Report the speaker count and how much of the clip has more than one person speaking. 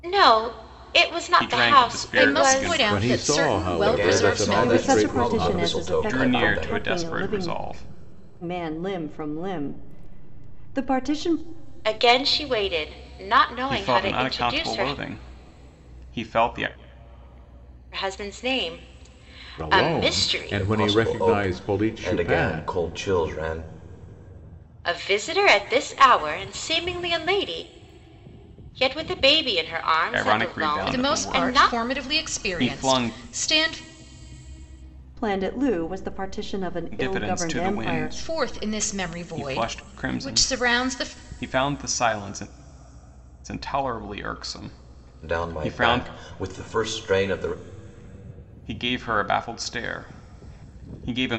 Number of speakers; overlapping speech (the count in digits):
6, about 37%